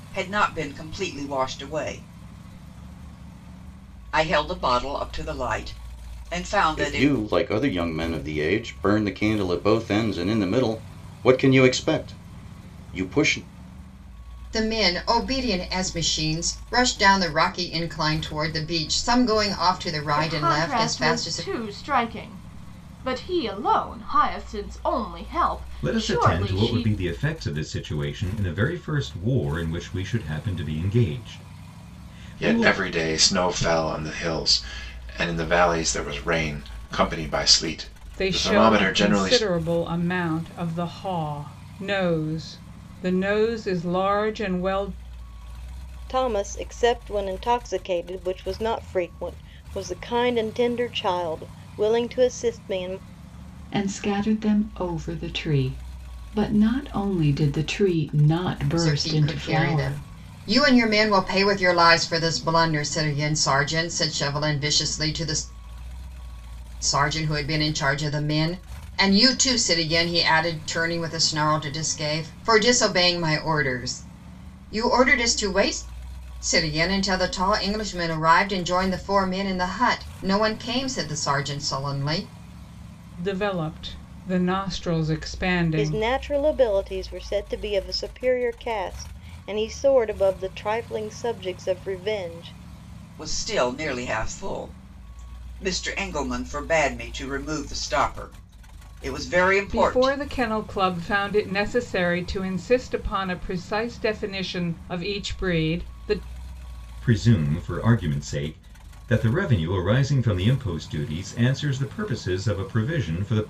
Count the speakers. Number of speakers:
nine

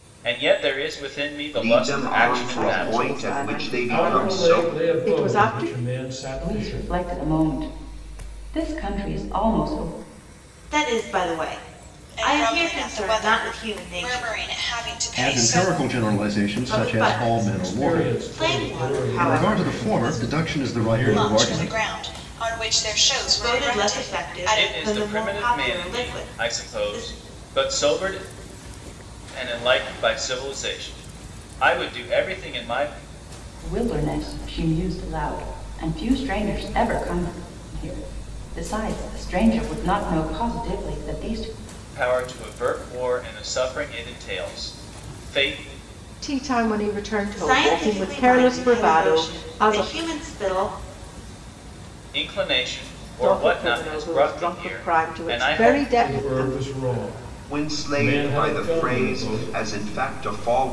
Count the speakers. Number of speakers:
eight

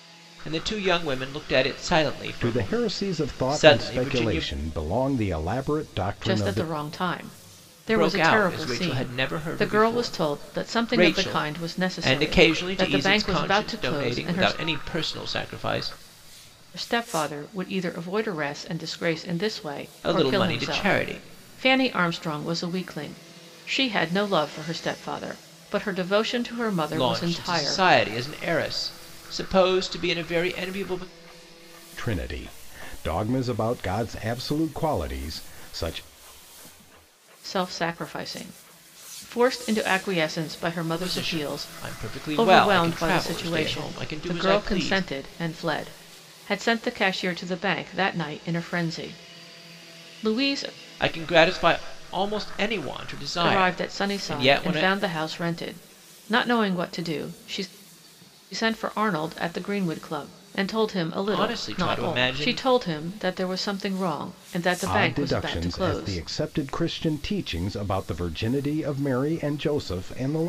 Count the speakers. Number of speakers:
three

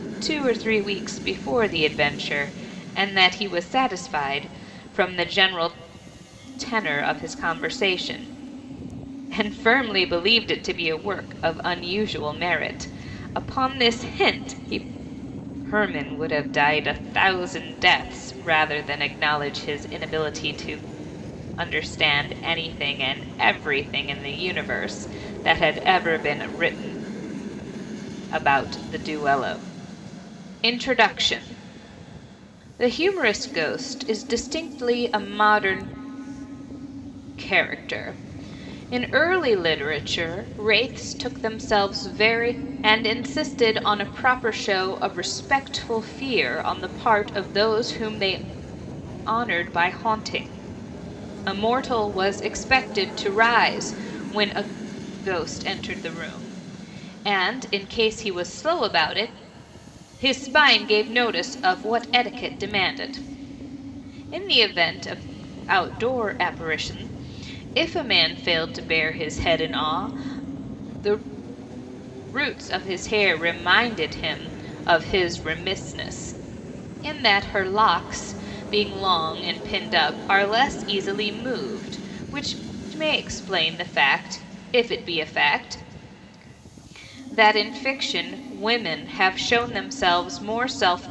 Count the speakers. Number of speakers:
one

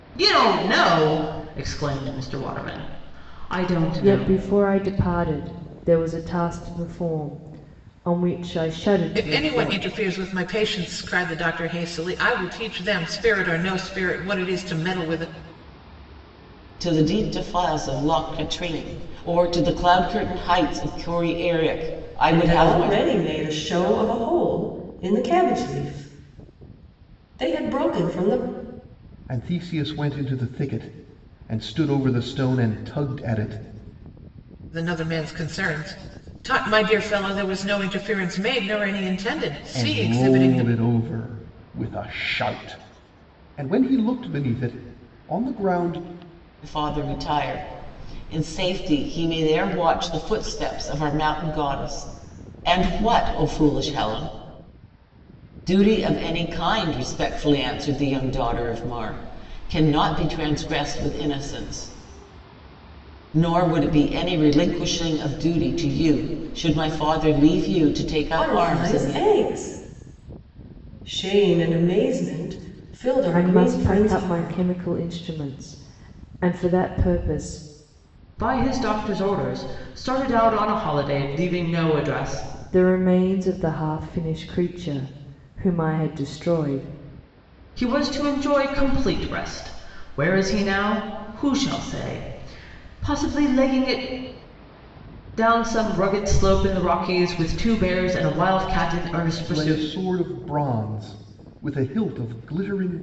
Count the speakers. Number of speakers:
six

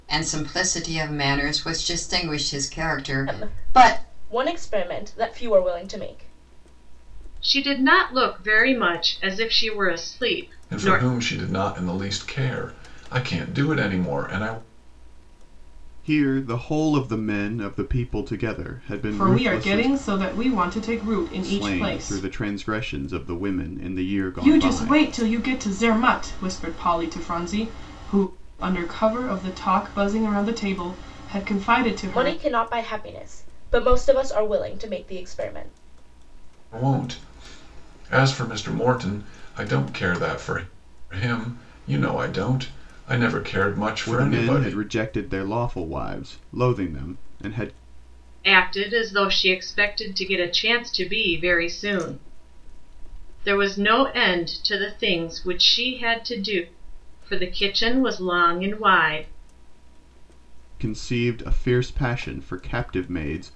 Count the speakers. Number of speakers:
six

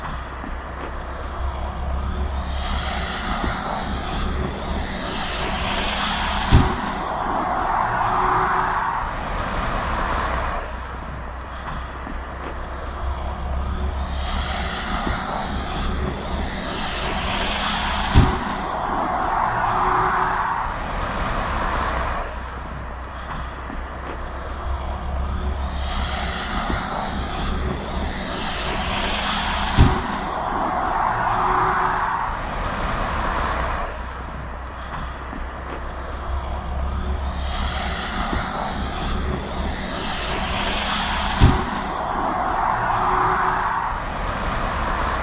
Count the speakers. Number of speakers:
zero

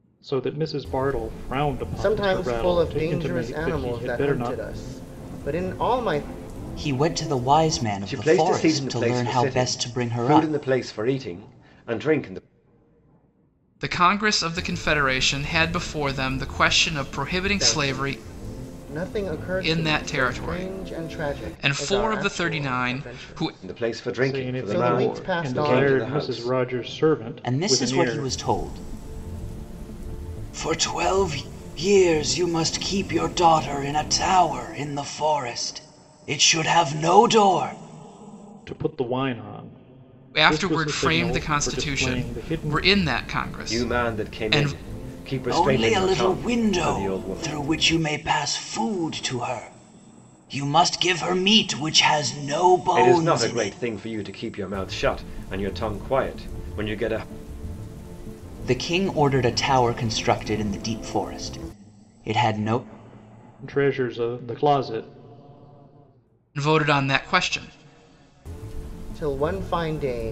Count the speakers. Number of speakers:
five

